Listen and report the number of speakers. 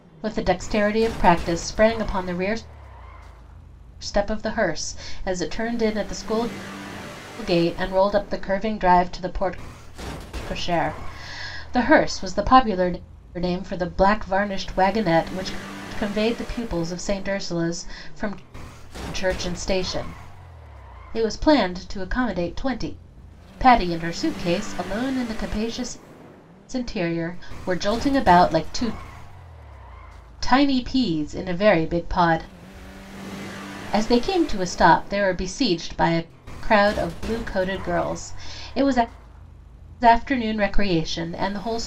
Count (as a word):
one